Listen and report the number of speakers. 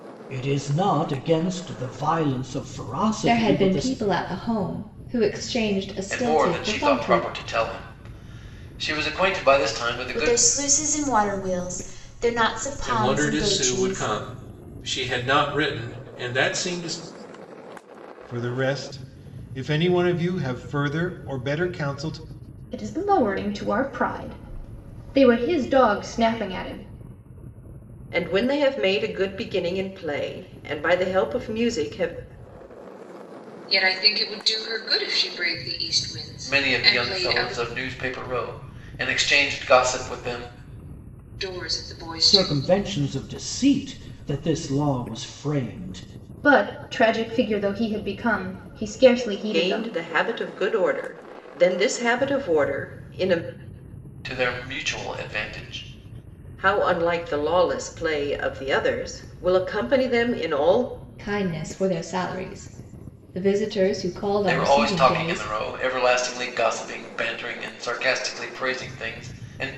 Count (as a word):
nine